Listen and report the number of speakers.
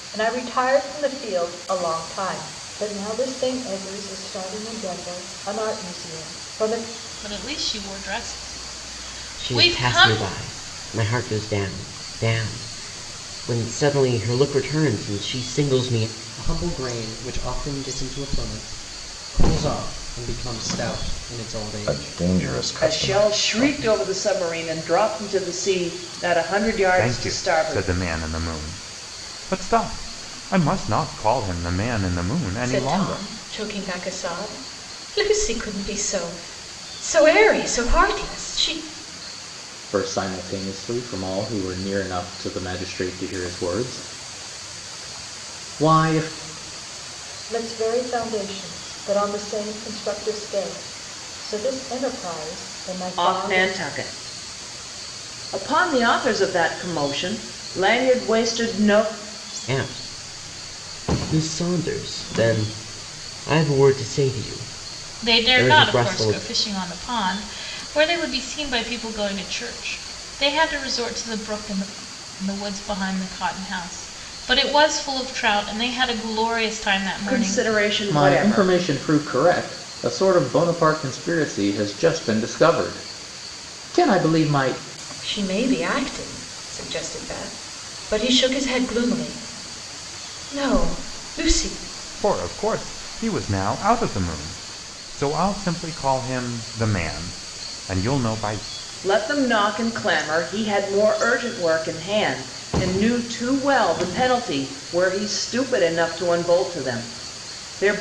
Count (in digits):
9